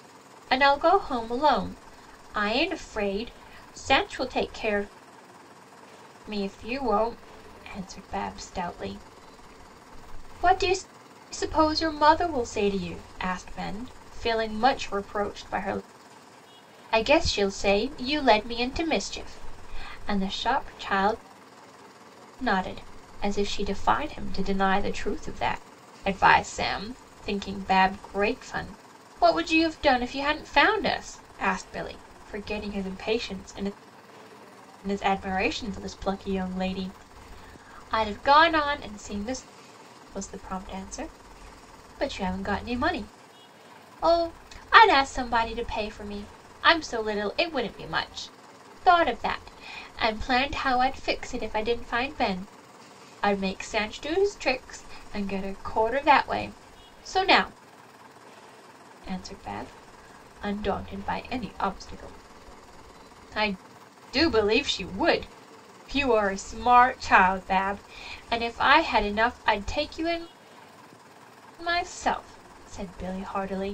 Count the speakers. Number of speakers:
one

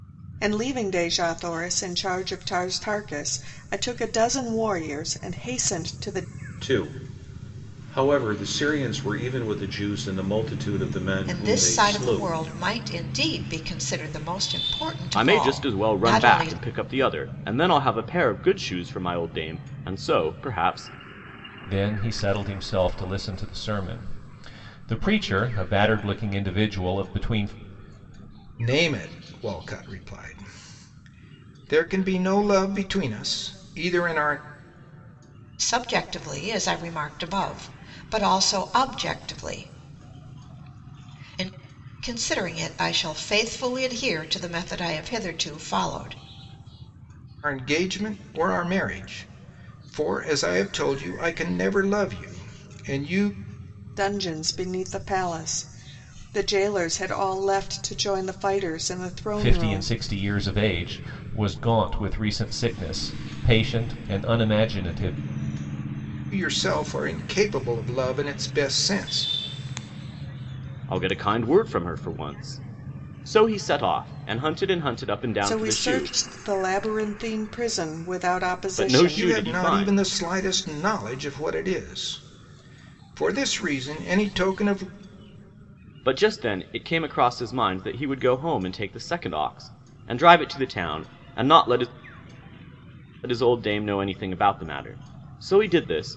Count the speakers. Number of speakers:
six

